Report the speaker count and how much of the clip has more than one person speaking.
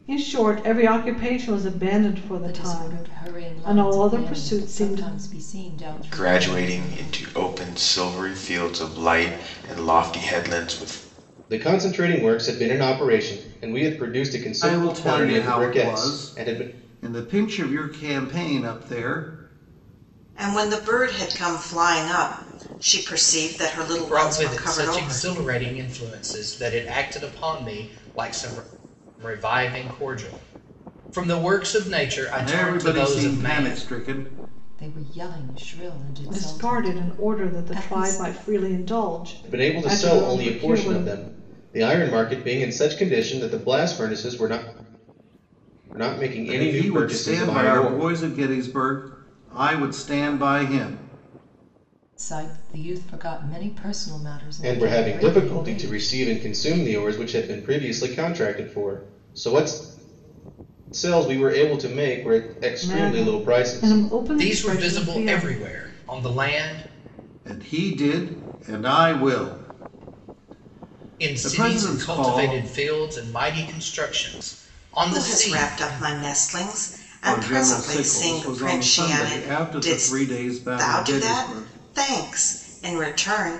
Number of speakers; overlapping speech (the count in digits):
7, about 31%